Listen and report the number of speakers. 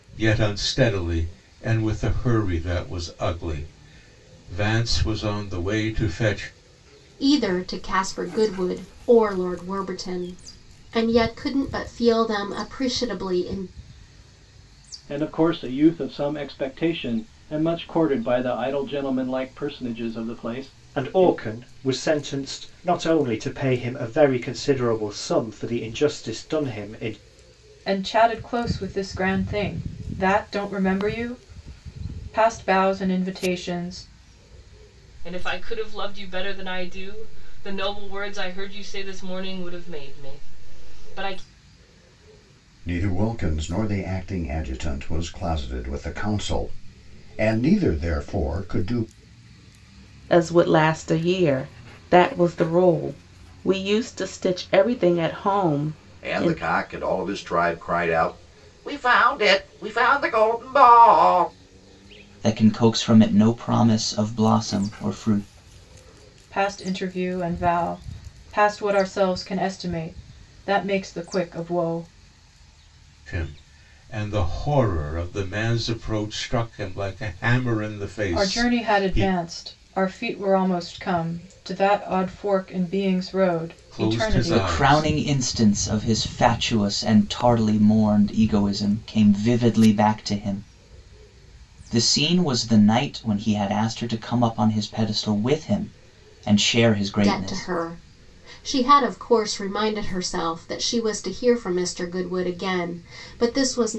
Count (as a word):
ten